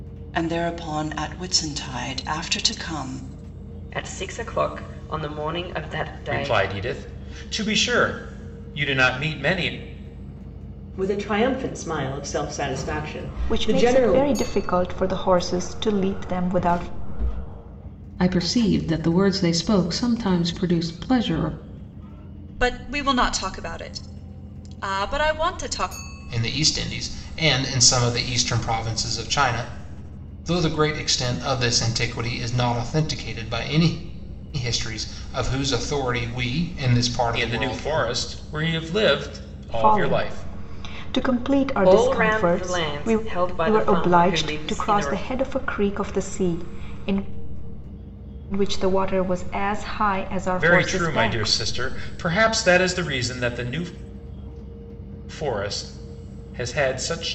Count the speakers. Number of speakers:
eight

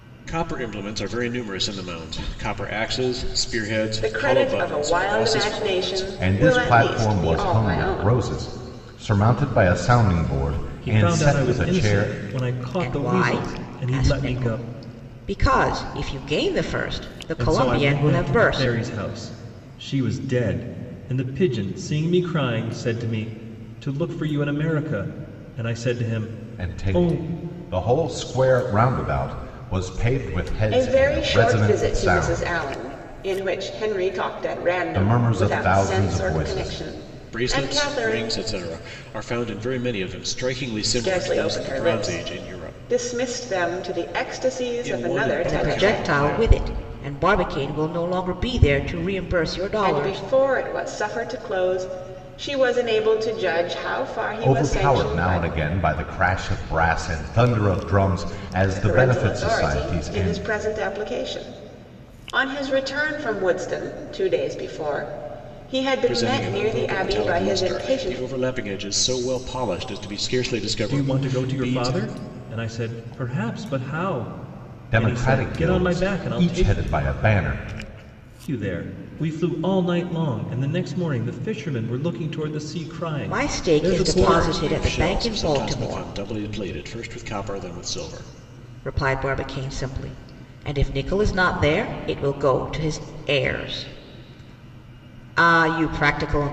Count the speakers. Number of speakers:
five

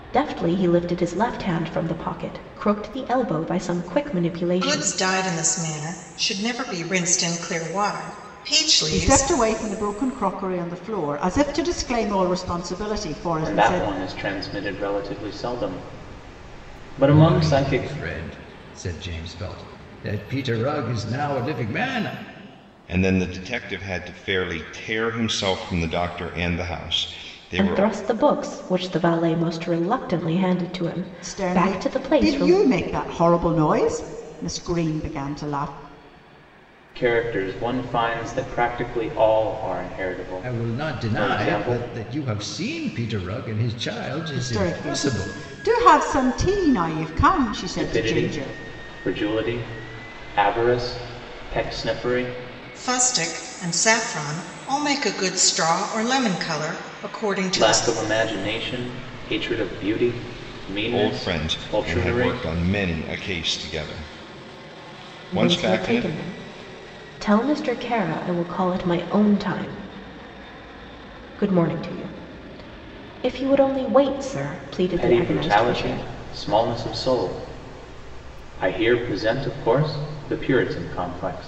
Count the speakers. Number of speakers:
six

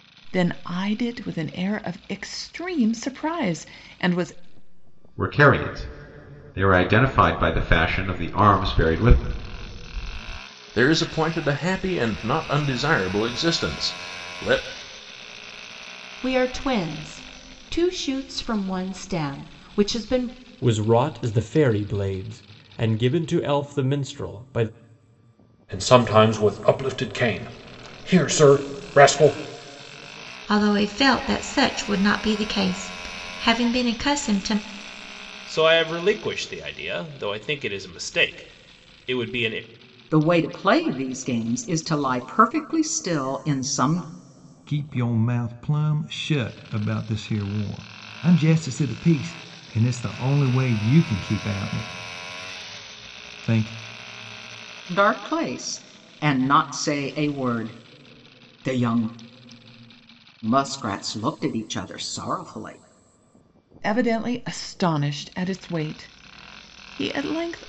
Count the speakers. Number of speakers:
ten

